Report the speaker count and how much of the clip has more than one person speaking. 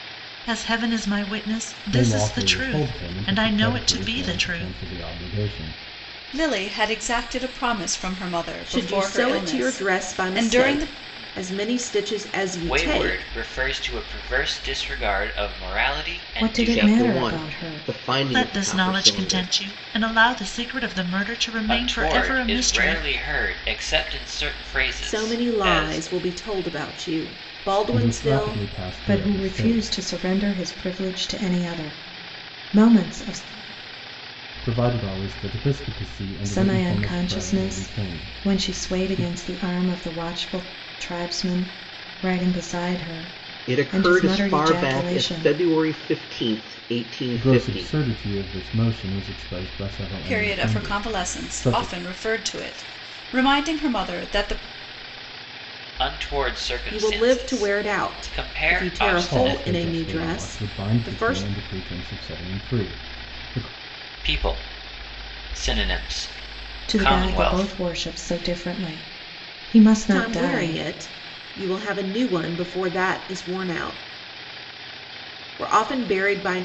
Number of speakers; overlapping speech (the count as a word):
seven, about 35%